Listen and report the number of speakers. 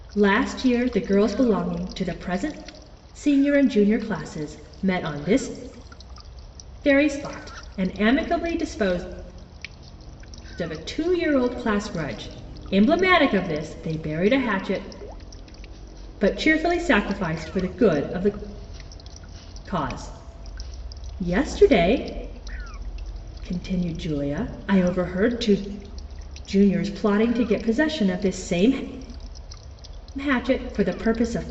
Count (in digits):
1